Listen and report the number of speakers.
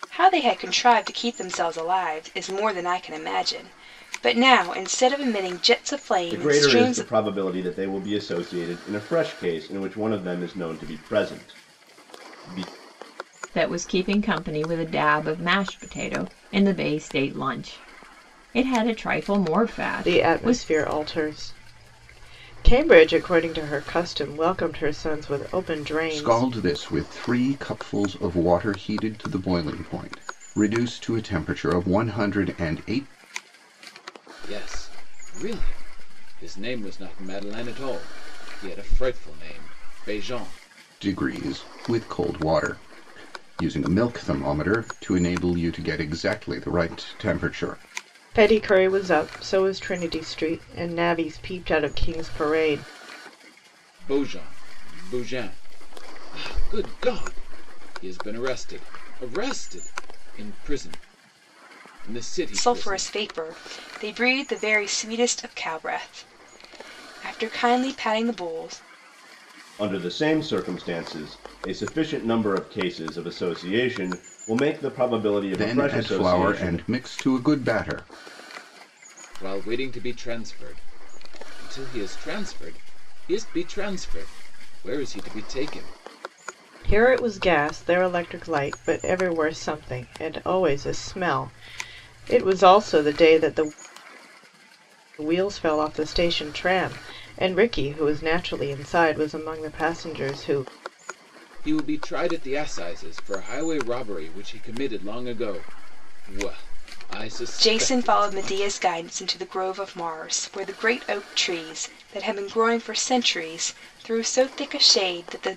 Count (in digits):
6